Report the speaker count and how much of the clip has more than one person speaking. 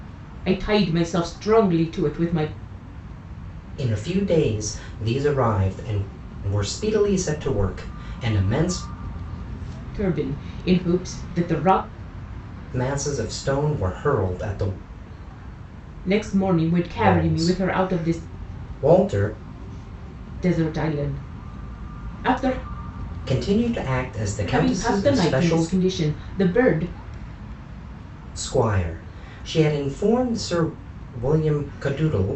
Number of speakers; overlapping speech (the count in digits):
2, about 8%